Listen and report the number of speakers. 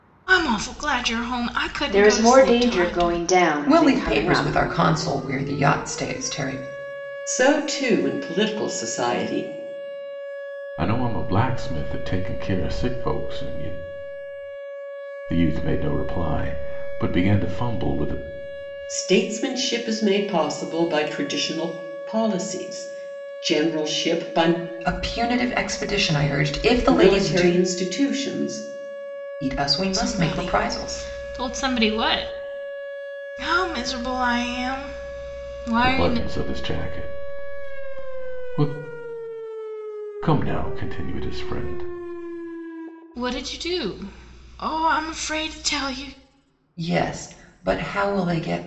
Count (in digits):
5